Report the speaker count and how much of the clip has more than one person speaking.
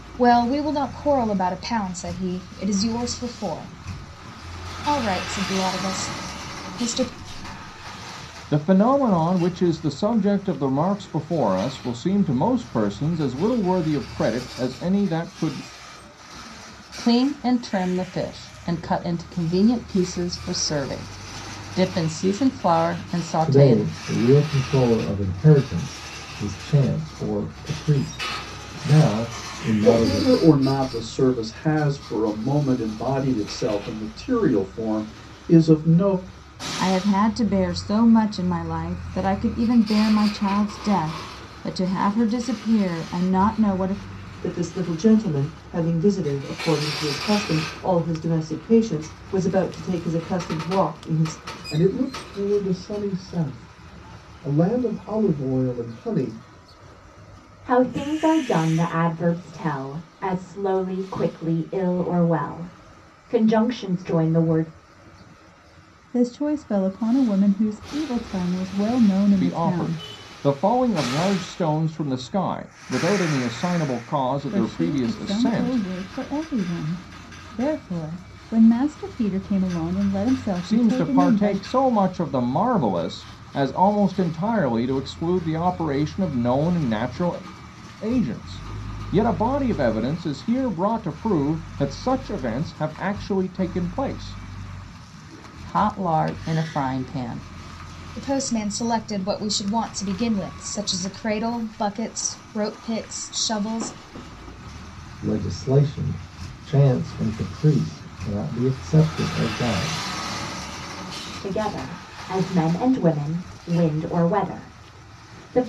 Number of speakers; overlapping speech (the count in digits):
10, about 4%